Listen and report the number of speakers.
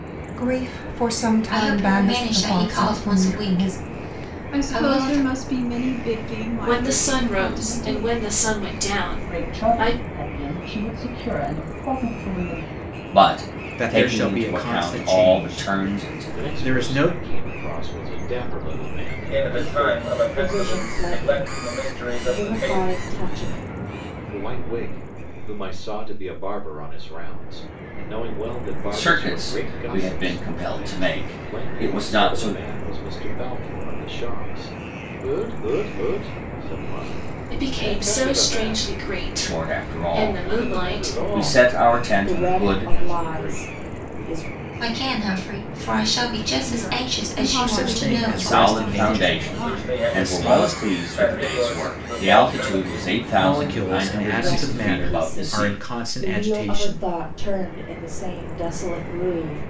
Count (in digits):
10